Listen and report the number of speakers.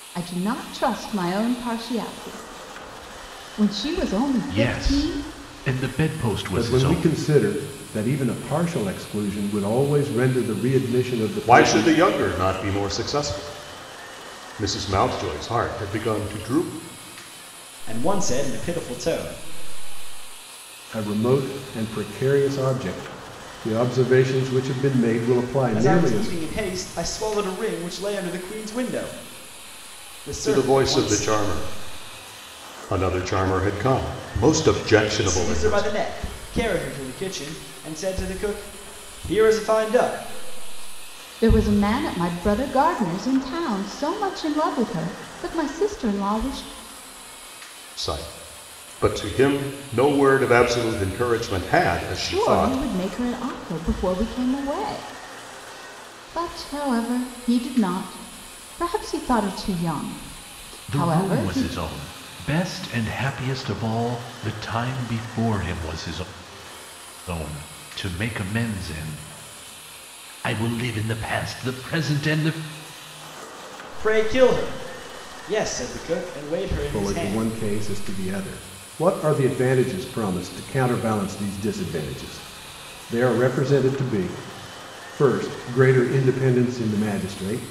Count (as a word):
five